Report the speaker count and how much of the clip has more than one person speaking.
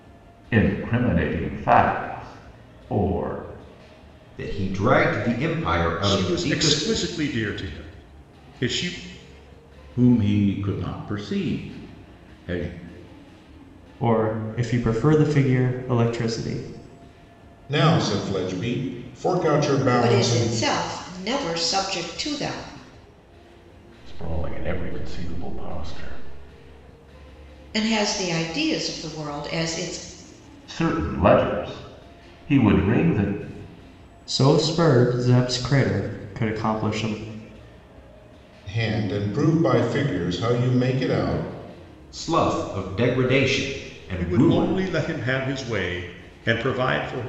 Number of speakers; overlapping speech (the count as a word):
eight, about 4%